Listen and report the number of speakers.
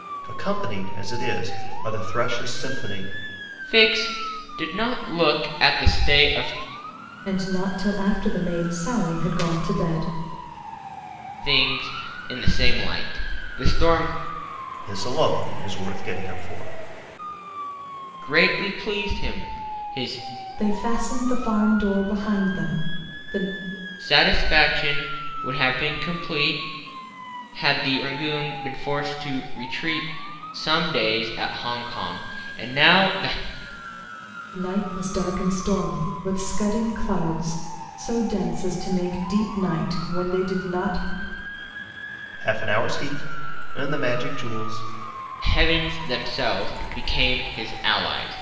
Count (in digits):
3